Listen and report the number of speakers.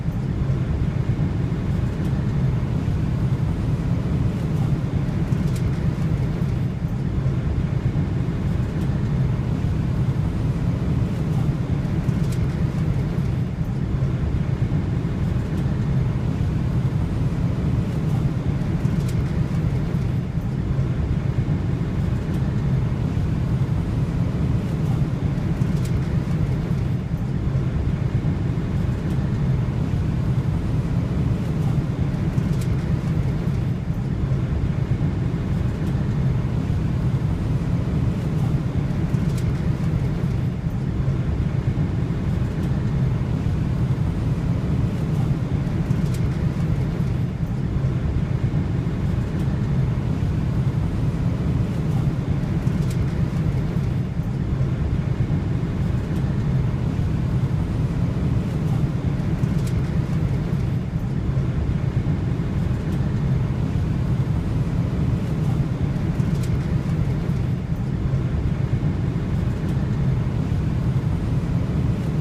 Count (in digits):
0